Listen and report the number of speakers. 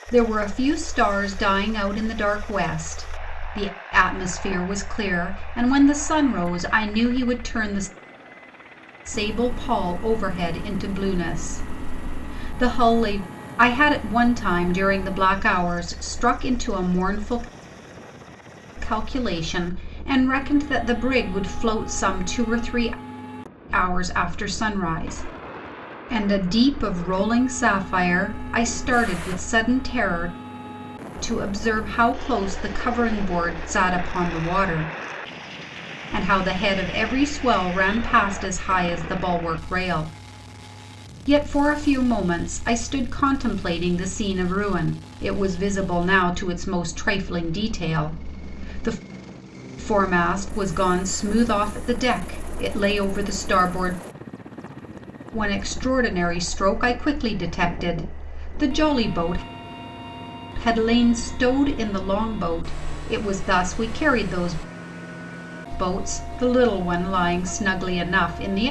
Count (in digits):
1